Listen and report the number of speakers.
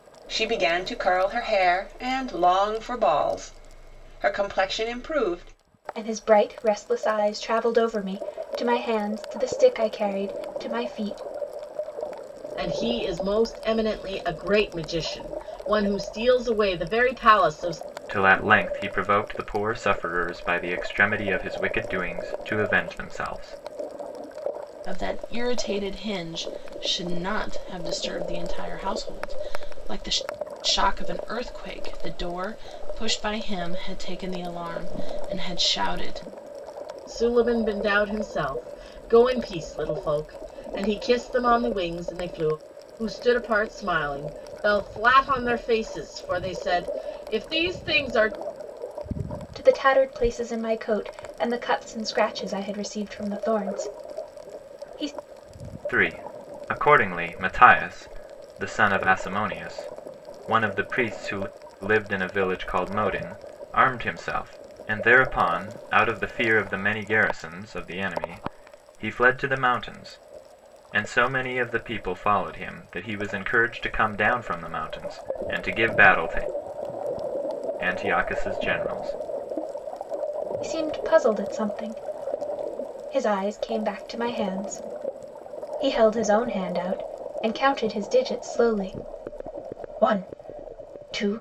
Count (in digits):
5